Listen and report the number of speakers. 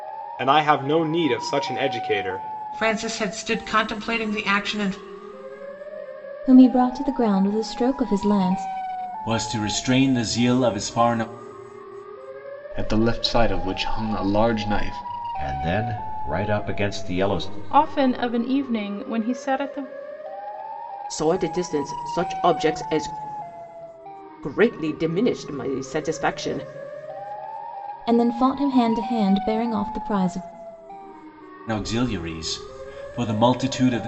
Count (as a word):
eight